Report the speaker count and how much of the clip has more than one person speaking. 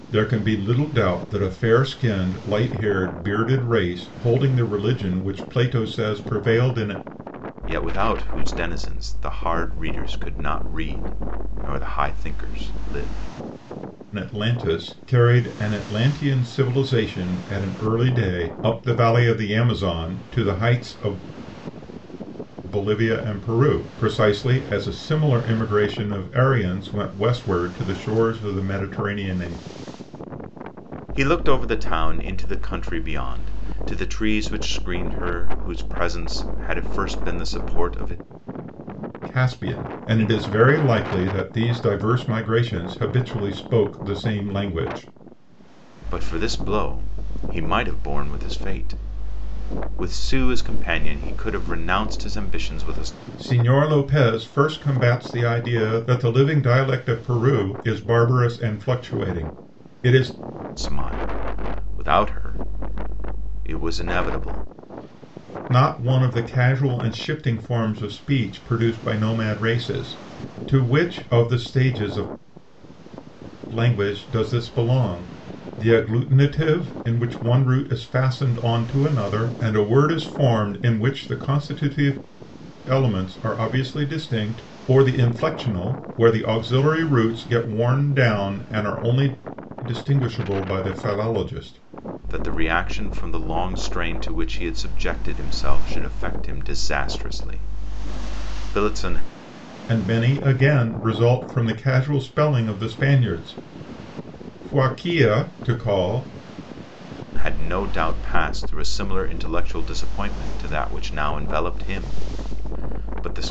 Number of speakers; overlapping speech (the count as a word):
two, no overlap